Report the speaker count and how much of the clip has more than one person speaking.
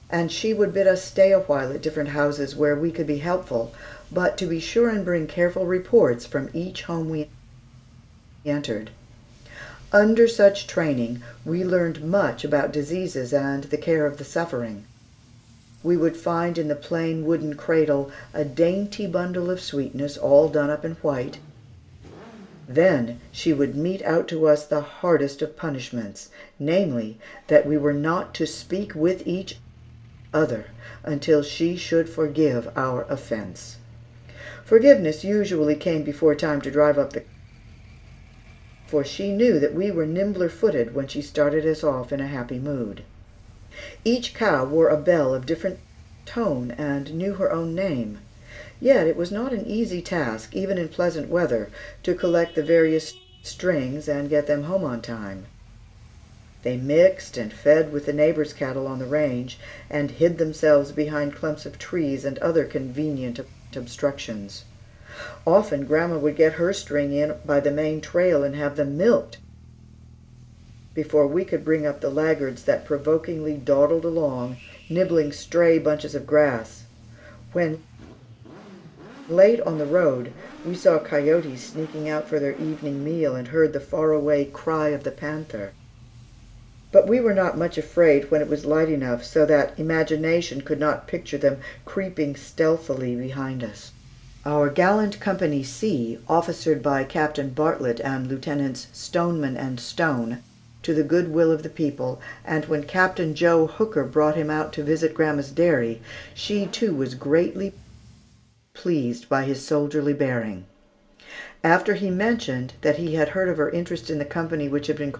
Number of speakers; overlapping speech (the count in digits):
1, no overlap